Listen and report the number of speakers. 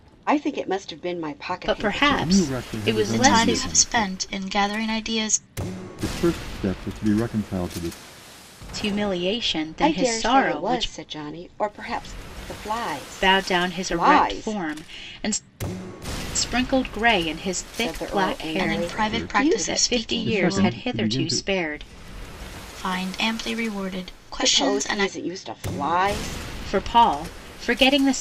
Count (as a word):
four